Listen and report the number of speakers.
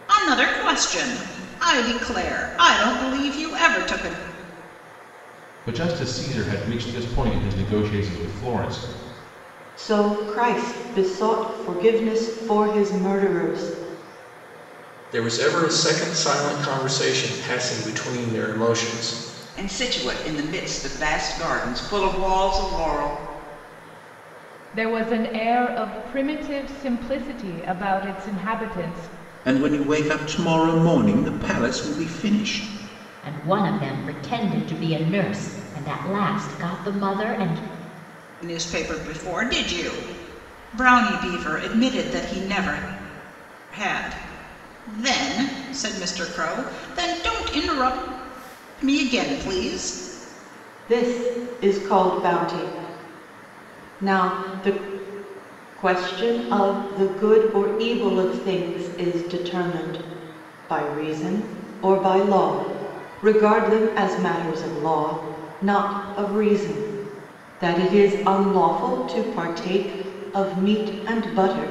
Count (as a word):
eight